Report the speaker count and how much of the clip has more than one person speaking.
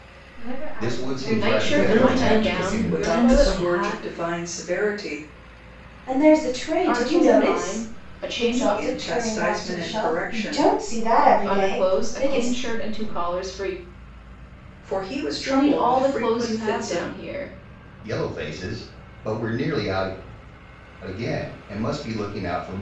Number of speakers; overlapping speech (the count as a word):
six, about 50%